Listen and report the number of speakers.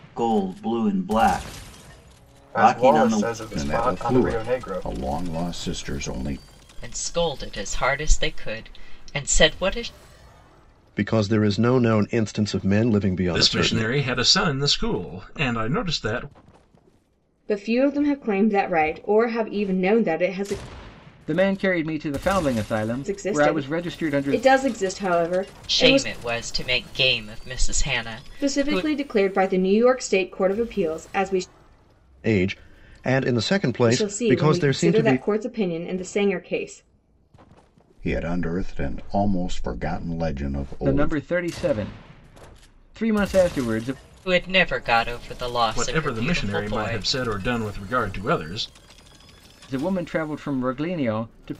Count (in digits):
8